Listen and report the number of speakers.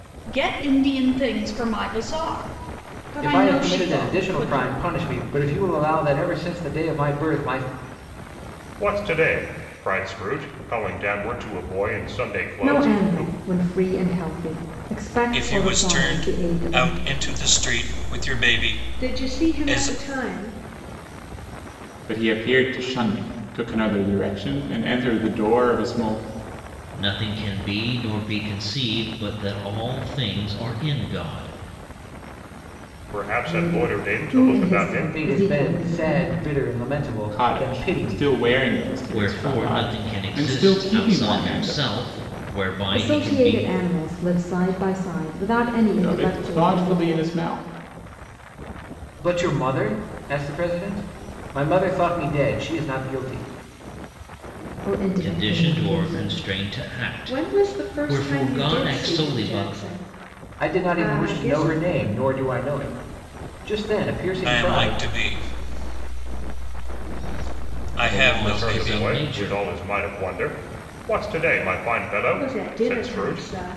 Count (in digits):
8